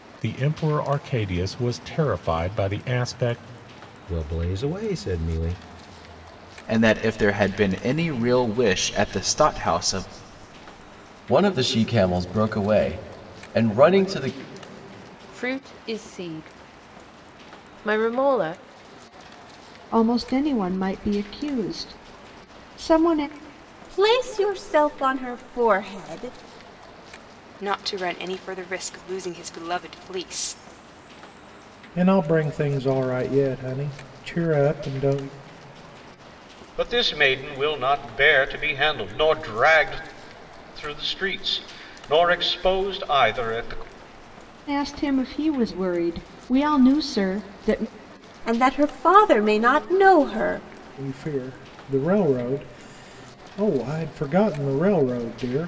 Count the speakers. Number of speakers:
ten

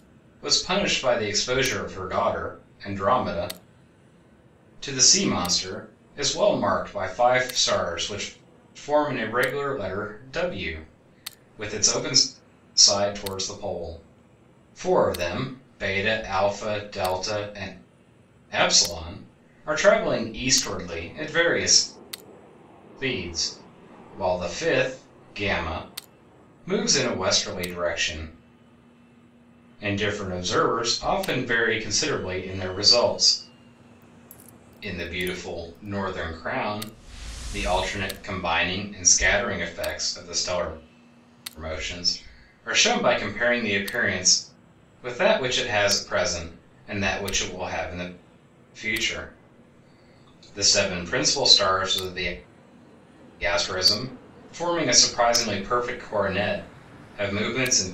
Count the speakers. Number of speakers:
one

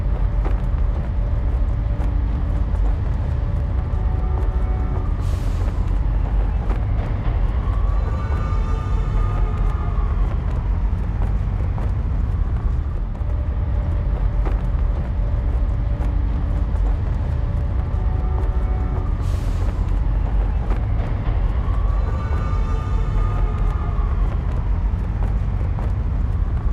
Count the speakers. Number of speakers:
zero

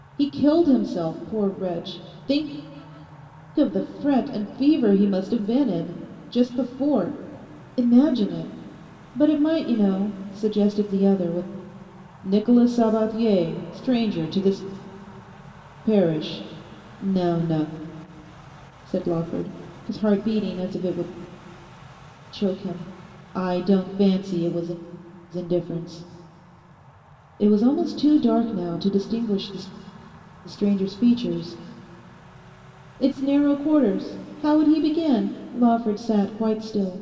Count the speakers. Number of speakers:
one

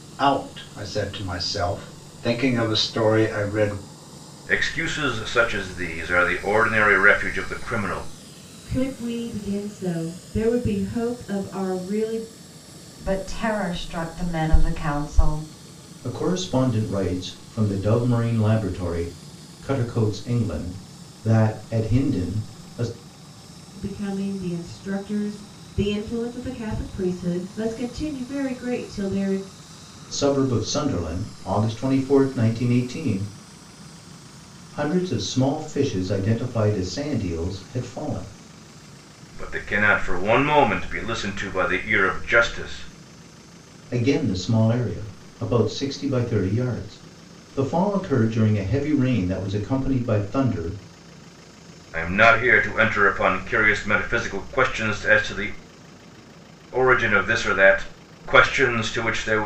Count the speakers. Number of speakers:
five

